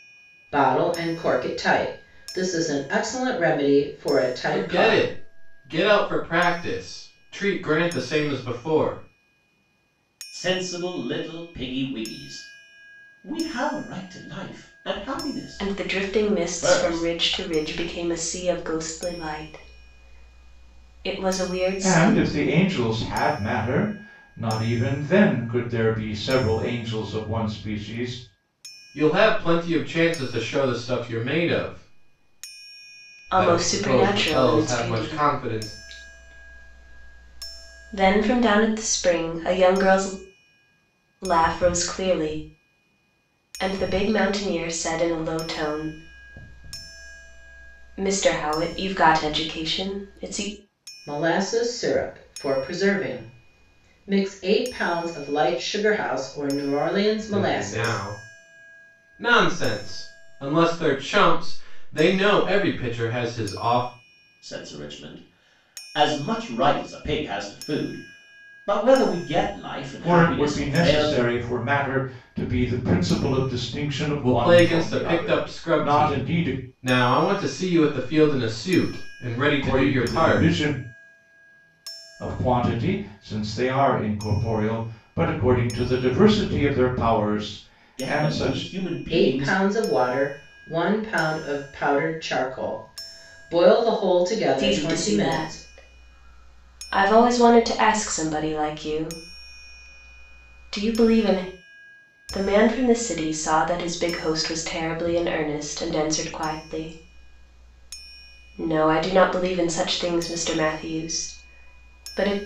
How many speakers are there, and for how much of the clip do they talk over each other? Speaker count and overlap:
5, about 12%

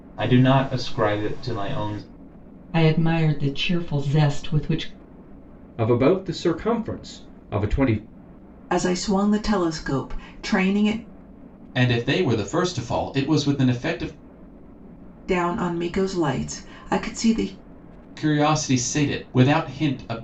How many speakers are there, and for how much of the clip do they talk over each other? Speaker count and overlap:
5, no overlap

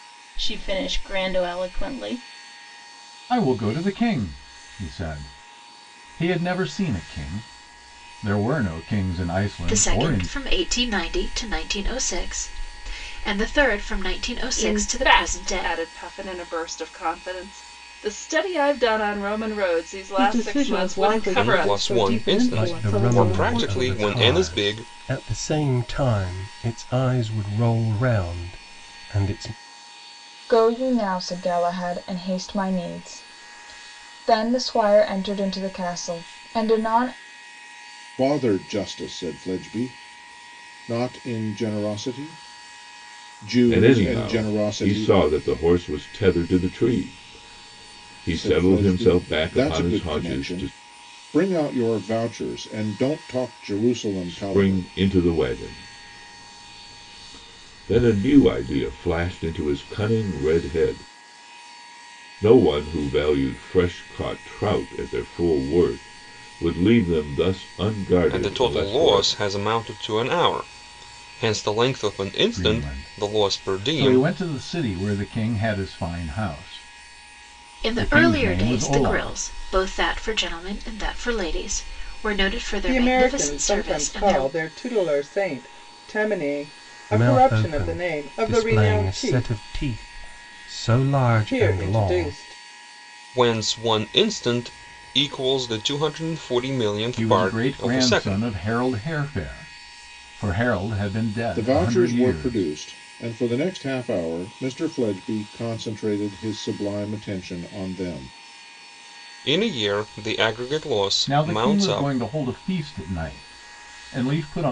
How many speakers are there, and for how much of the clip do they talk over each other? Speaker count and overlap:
10, about 21%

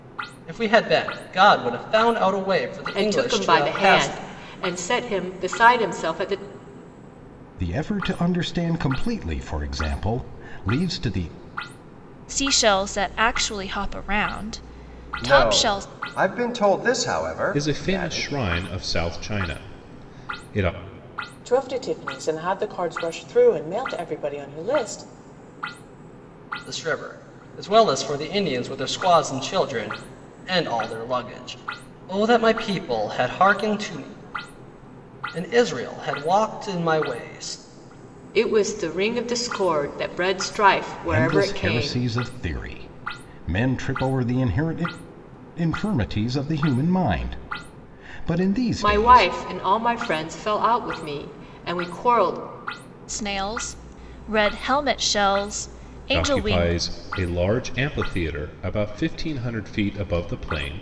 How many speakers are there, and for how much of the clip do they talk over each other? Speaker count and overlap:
7, about 8%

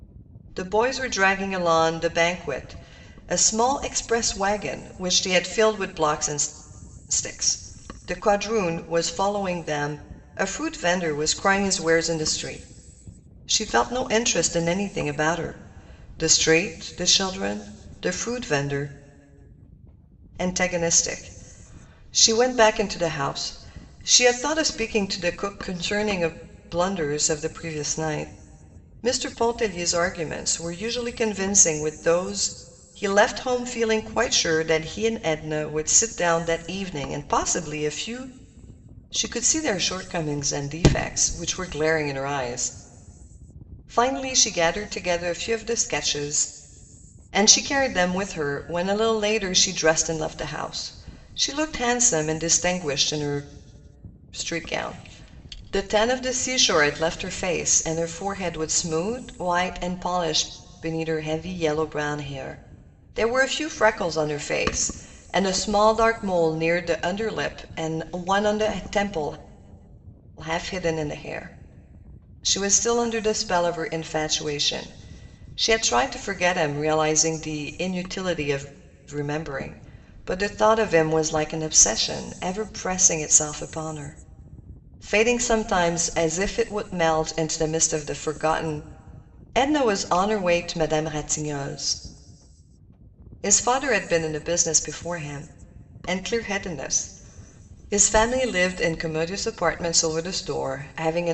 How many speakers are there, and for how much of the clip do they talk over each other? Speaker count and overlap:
1, no overlap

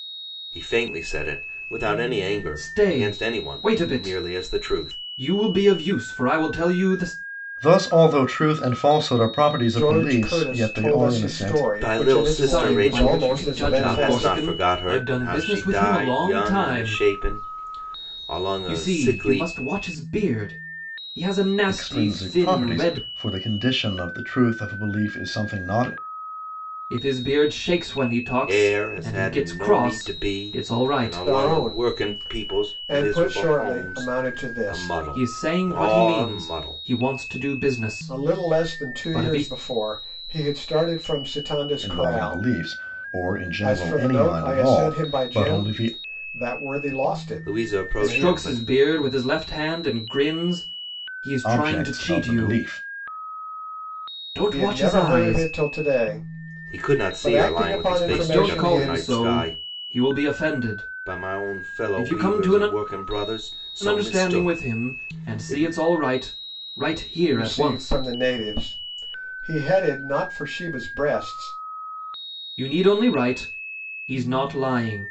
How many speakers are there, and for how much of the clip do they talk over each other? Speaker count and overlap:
4, about 47%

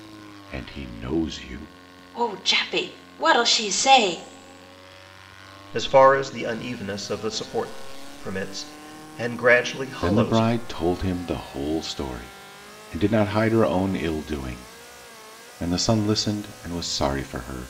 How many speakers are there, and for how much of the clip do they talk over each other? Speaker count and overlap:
3, about 3%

